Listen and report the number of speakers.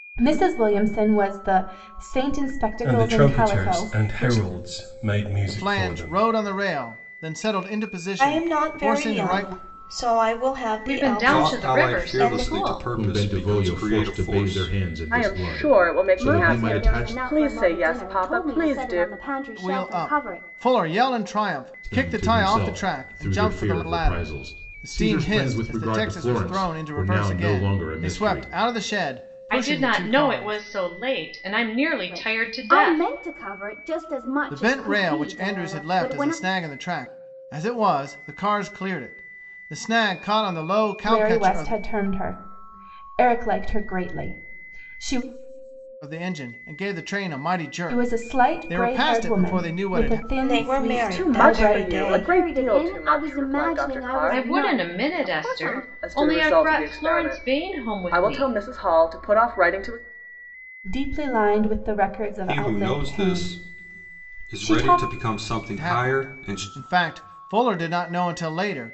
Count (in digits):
9